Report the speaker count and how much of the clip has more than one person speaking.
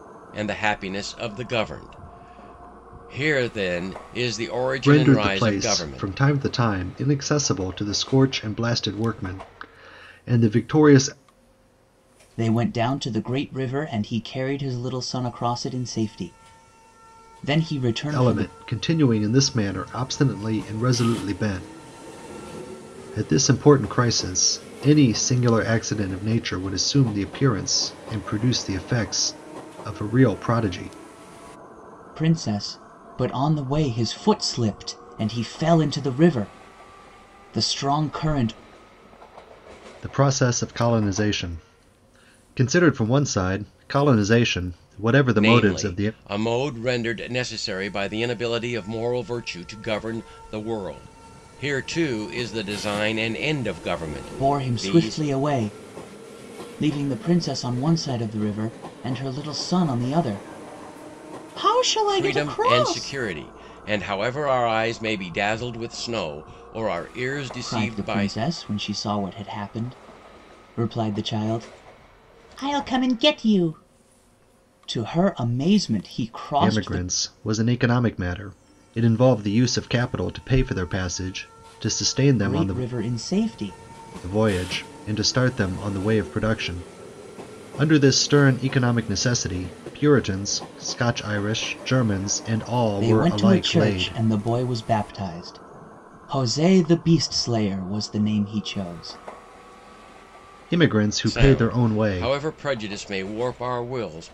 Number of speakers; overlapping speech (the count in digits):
3, about 8%